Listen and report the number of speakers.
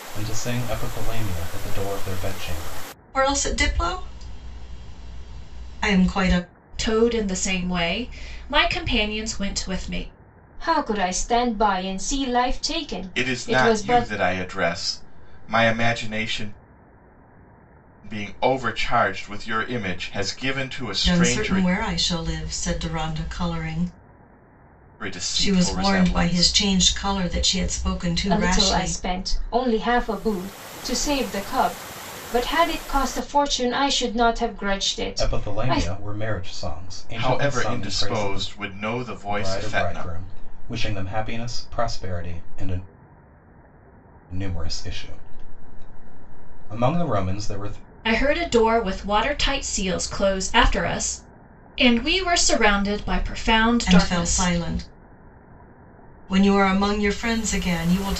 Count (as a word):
five